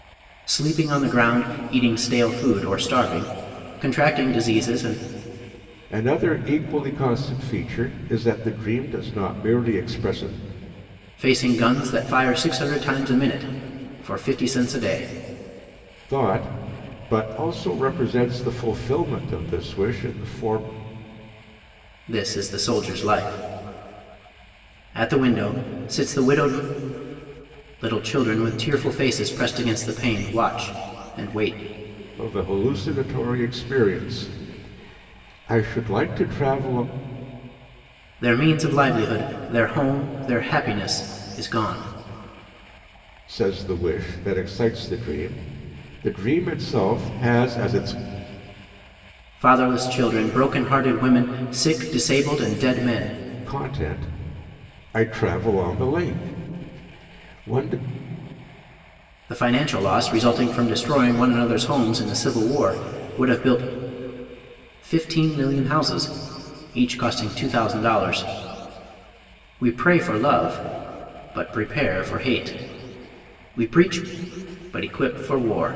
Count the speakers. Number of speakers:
2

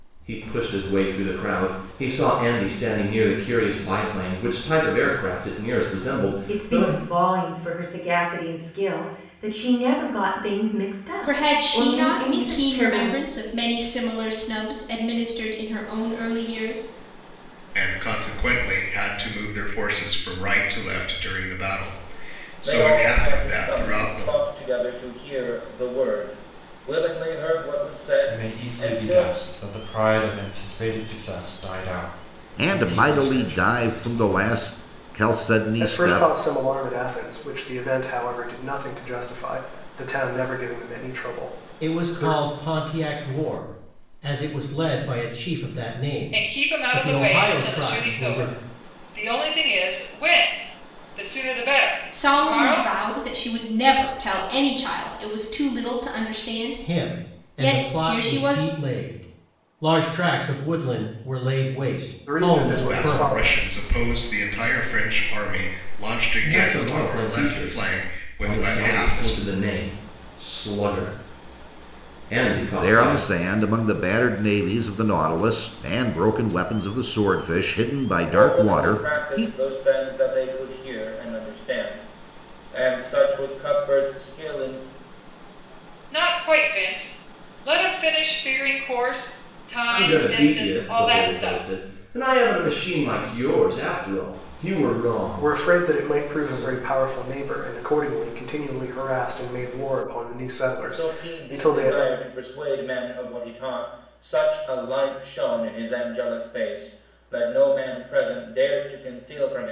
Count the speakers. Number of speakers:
10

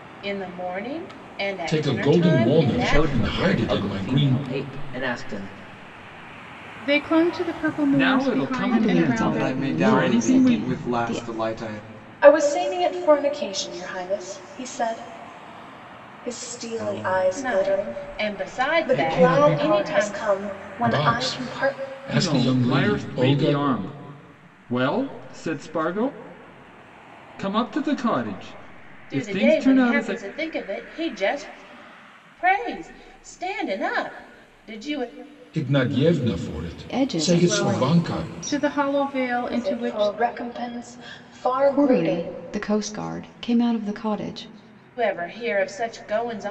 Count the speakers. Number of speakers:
8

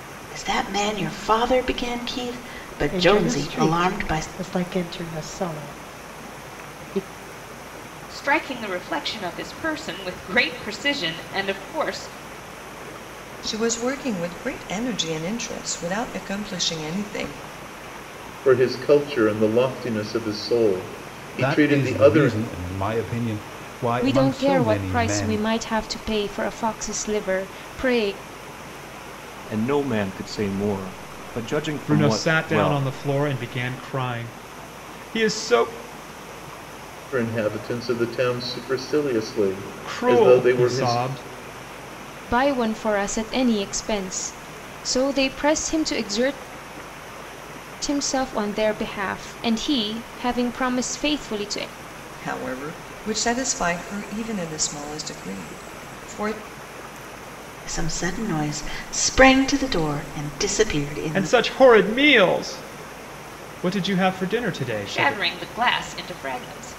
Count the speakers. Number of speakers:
9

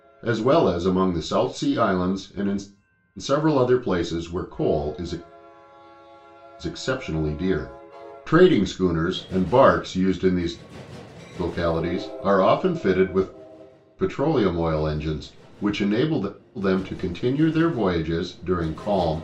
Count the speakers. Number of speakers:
1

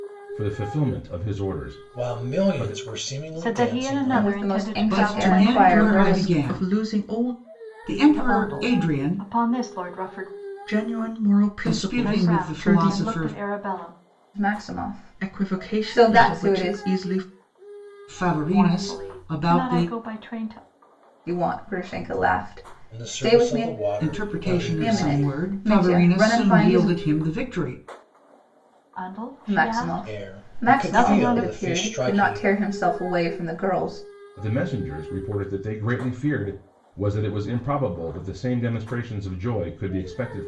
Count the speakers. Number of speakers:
6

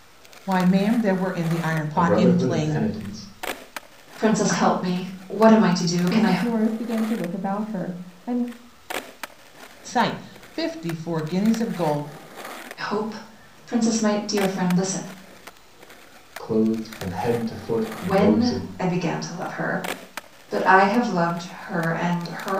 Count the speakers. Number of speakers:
4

